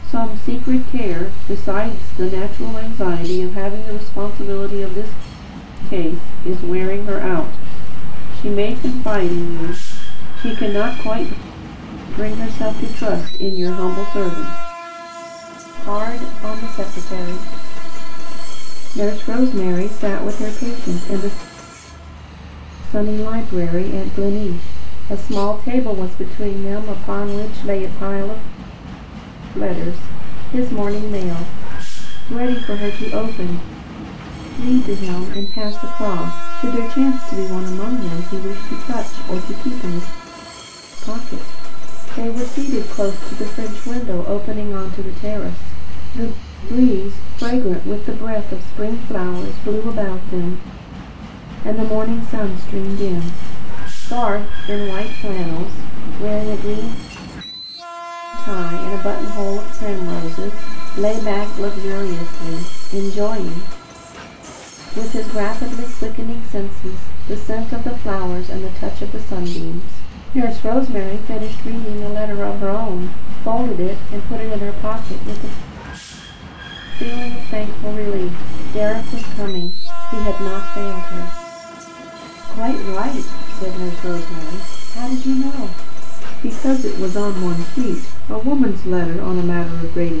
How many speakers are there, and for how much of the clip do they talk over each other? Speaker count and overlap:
1, no overlap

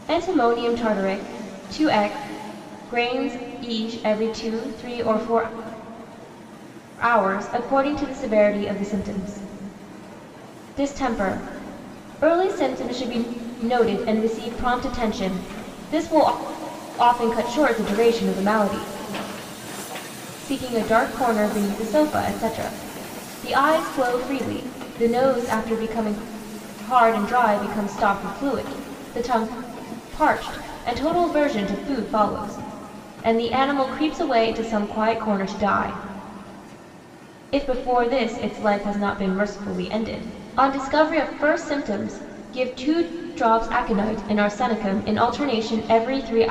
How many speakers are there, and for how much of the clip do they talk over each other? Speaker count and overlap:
1, no overlap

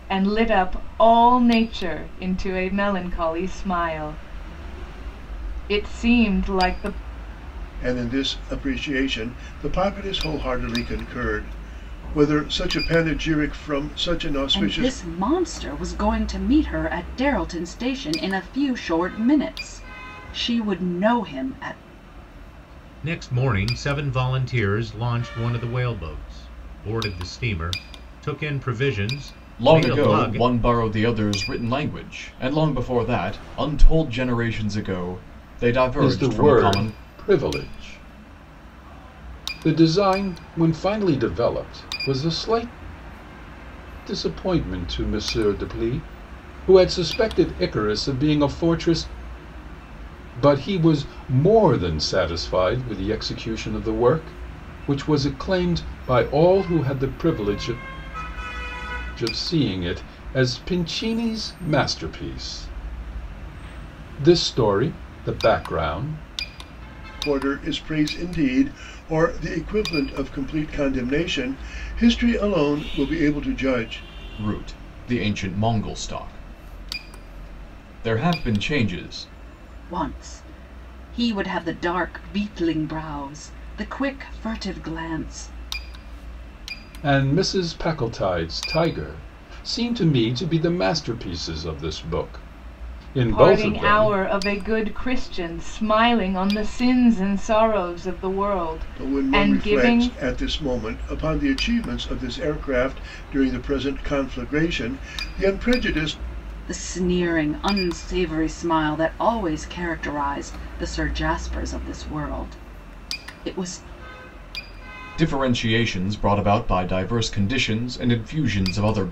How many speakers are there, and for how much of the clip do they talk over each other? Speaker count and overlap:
6, about 4%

